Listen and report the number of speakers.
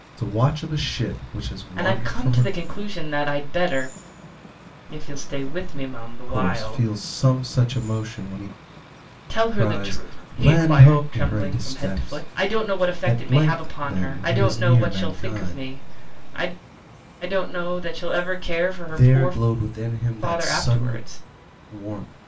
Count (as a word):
two